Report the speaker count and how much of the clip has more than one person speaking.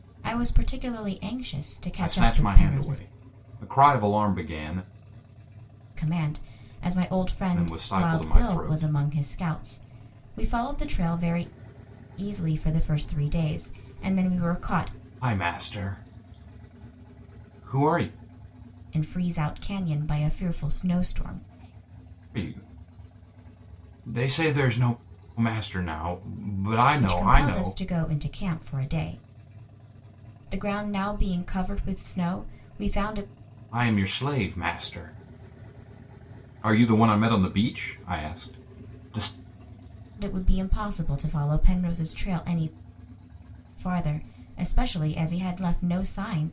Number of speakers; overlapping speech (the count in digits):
2, about 7%